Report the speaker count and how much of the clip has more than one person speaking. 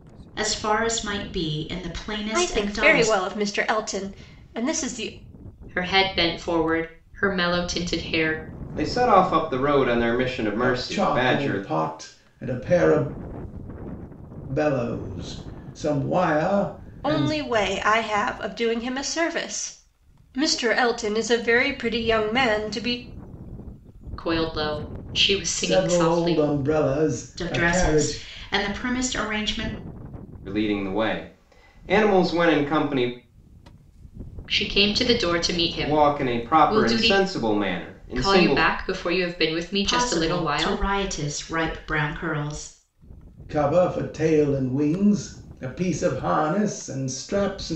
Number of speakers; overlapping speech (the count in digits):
5, about 15%